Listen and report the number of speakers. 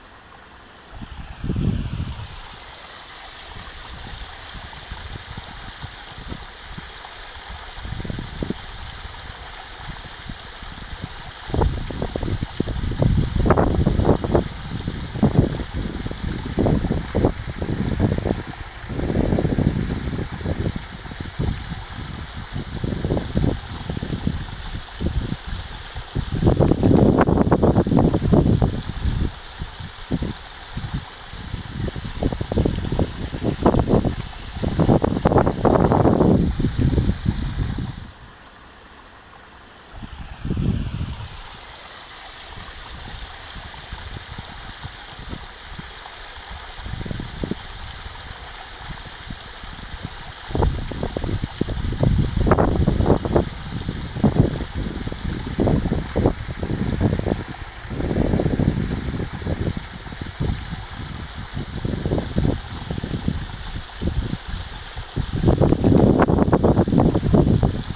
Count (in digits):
0